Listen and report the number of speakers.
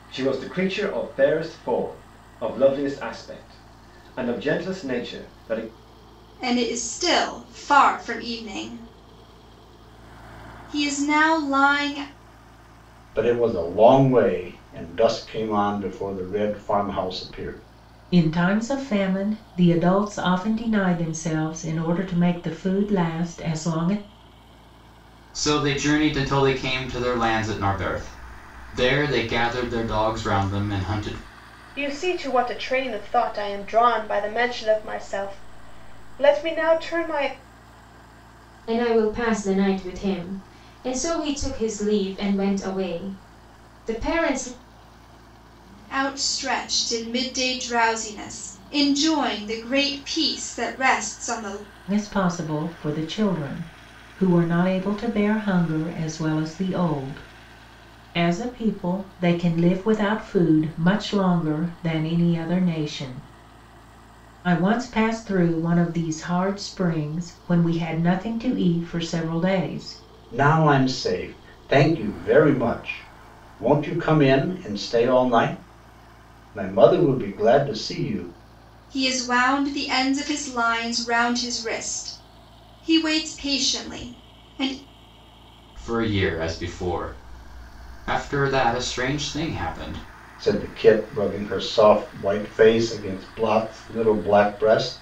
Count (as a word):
seven